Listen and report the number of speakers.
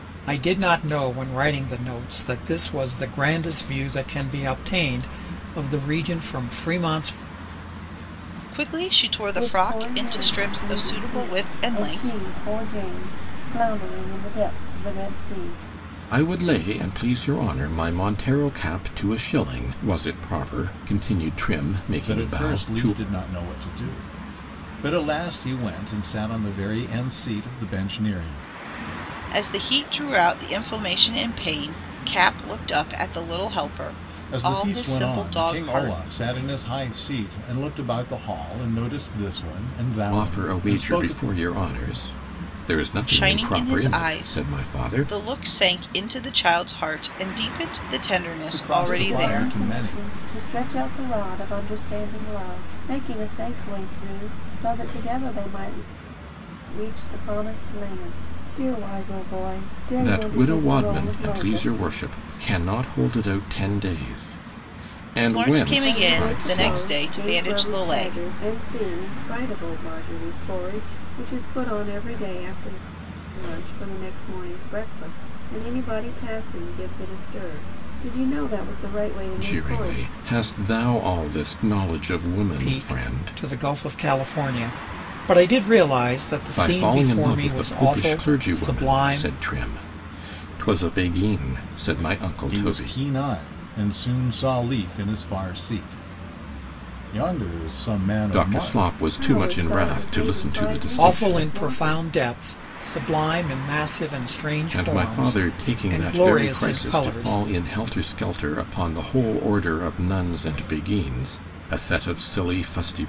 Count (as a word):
five